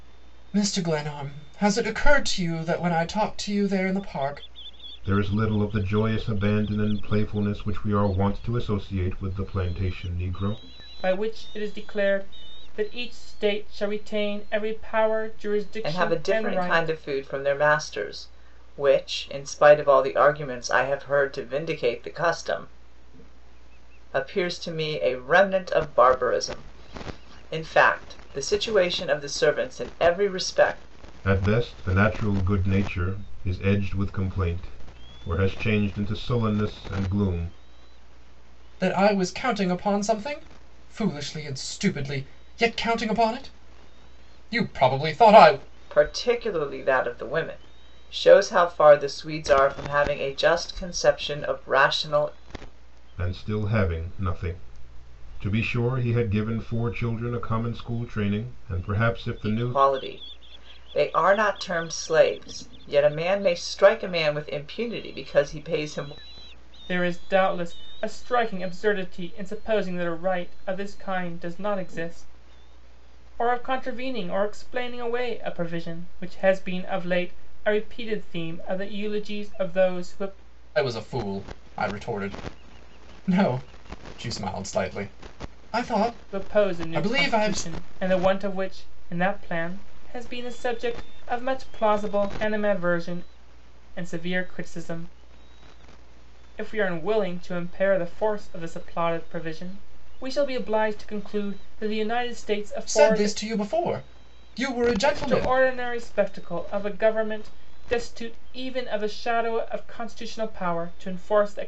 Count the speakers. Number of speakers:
four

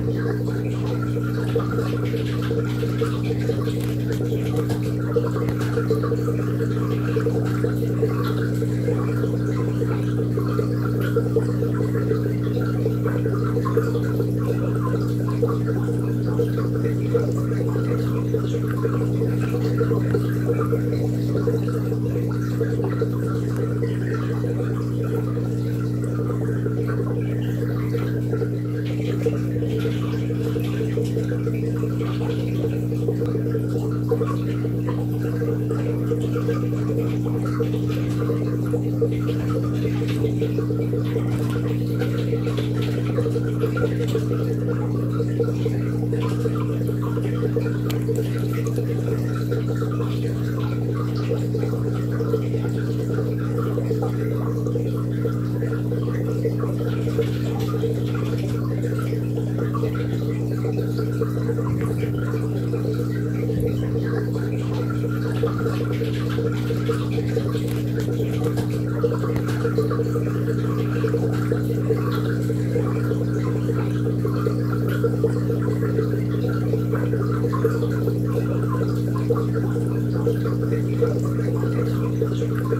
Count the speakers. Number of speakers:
zero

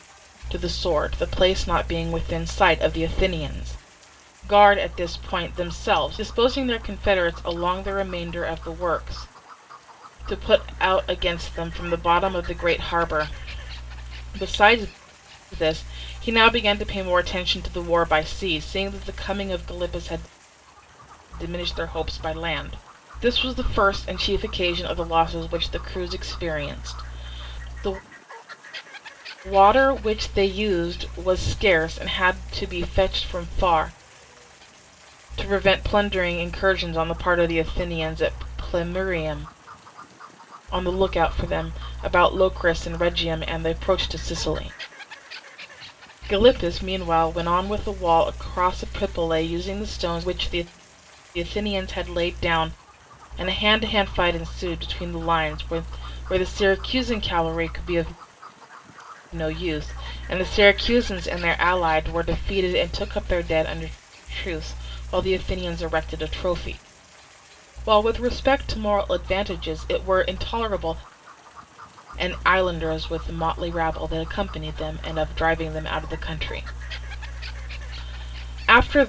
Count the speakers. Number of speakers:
one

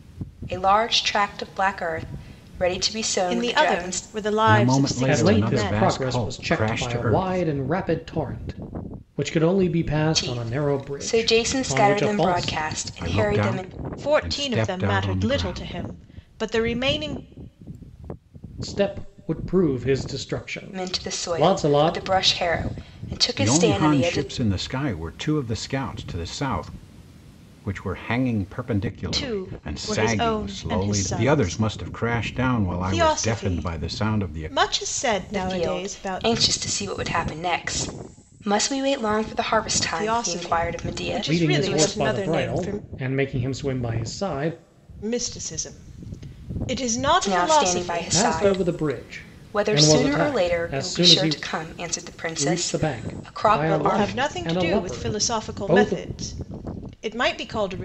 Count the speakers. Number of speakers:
four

